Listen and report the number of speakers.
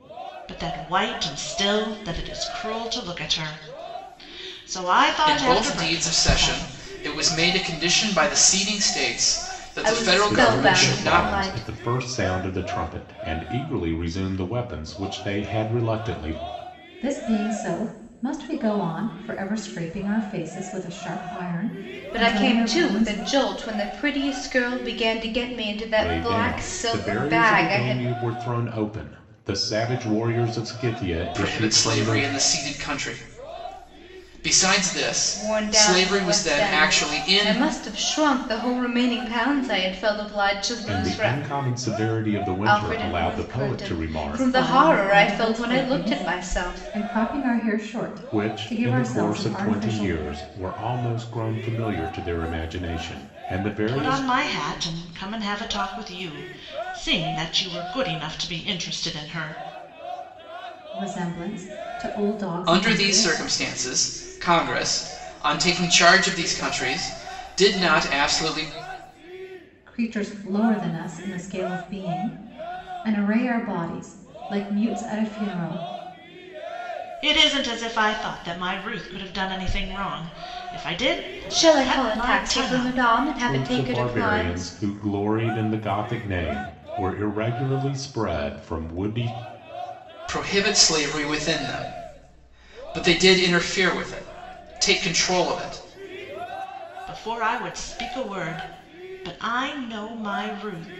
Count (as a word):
five